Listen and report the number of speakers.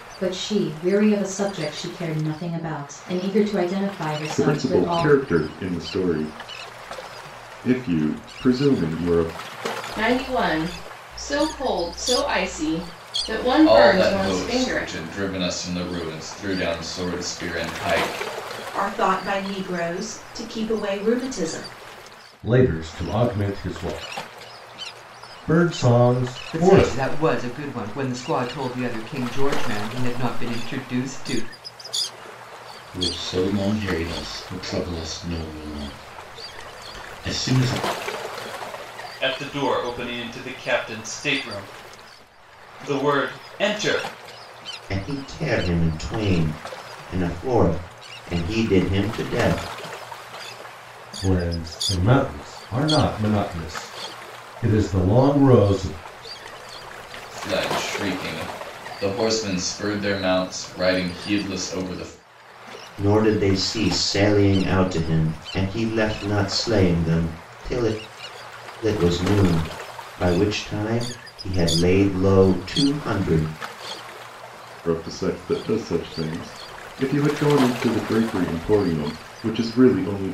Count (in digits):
10